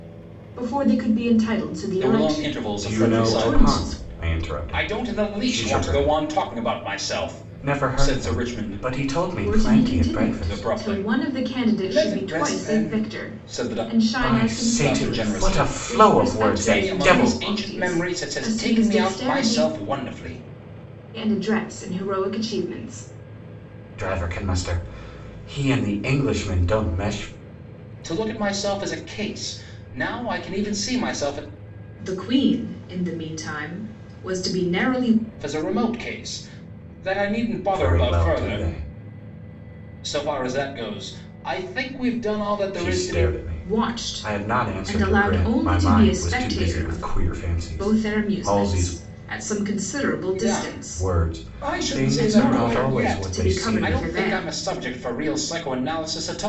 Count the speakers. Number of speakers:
3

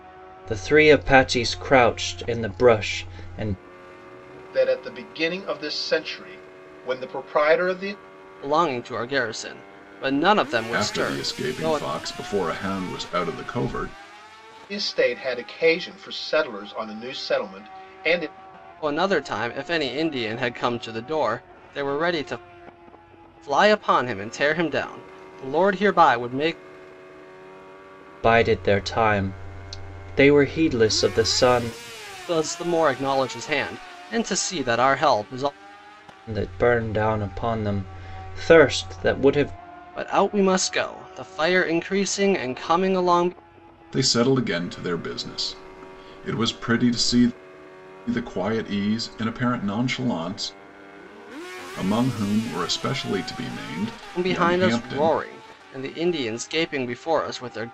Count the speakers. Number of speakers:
4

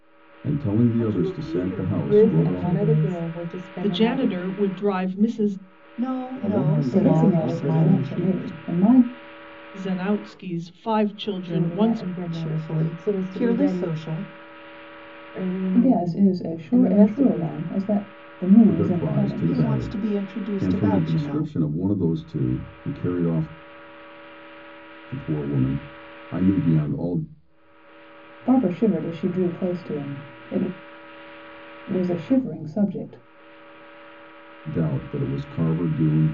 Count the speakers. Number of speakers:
7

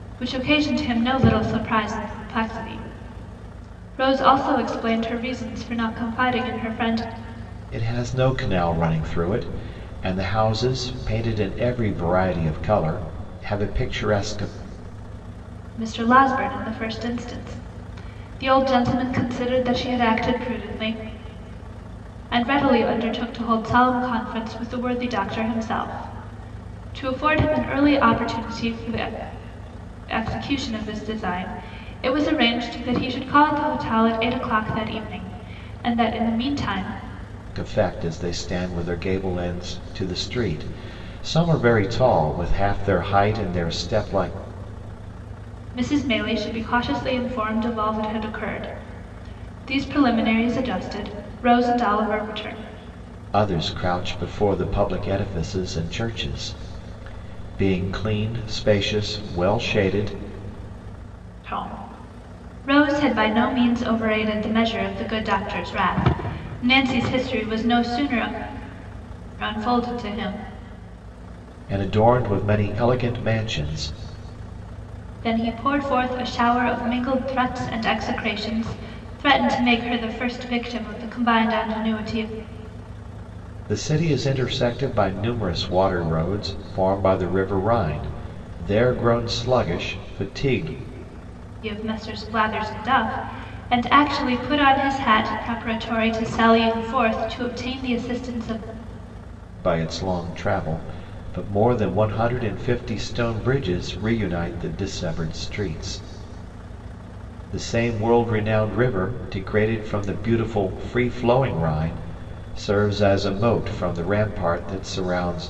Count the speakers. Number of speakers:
2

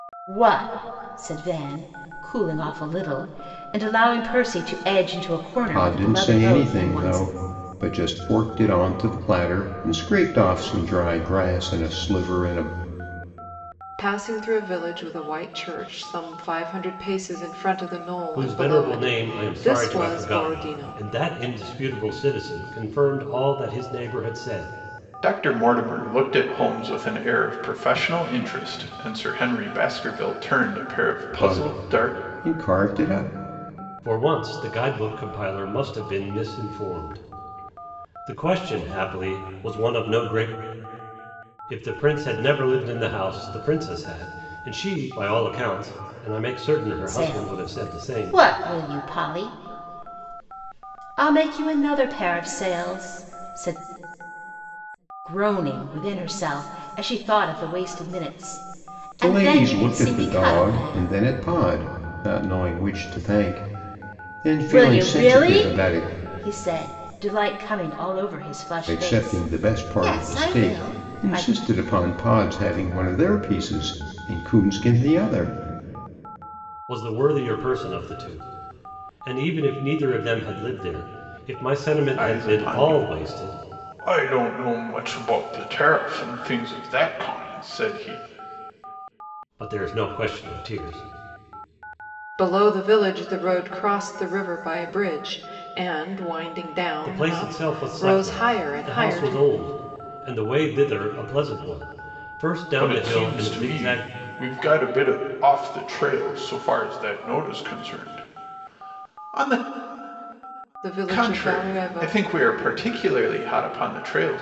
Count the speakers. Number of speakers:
5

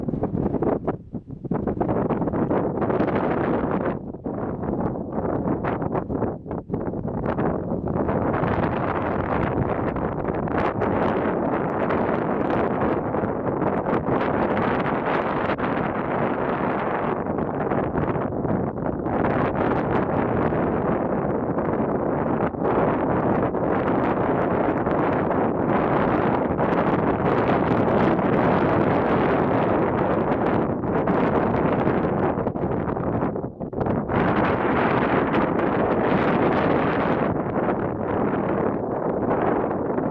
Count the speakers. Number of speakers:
0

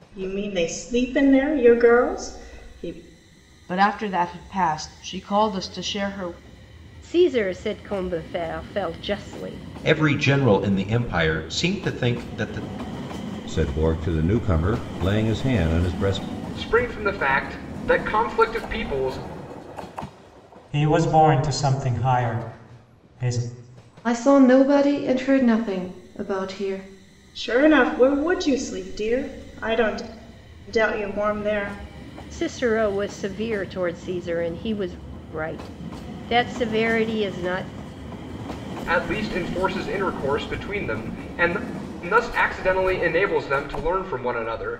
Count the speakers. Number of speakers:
8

